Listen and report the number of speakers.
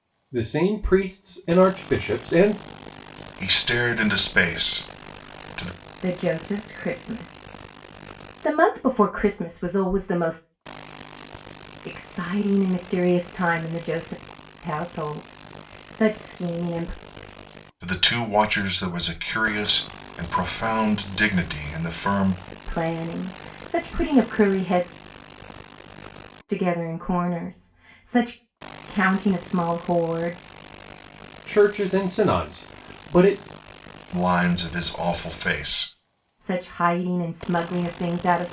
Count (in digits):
3